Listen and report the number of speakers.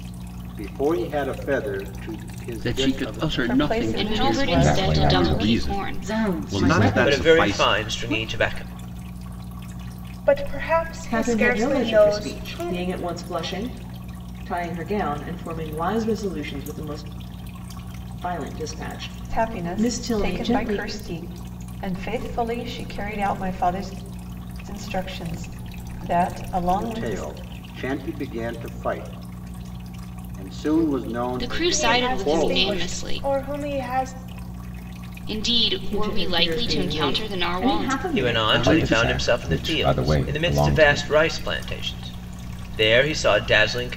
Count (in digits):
10